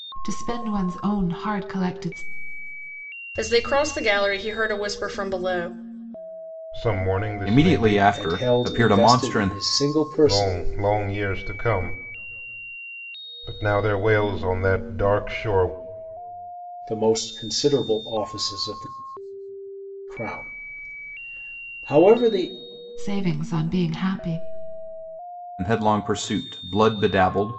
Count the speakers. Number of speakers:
5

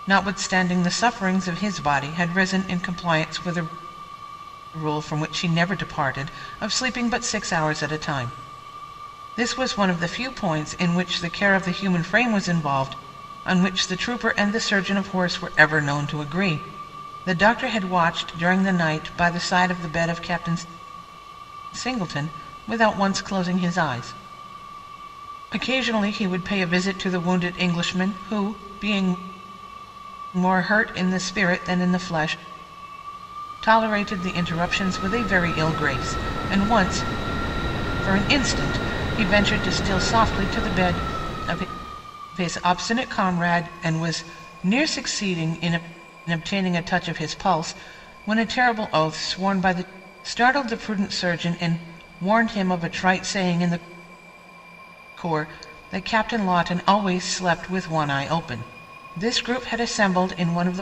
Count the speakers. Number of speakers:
1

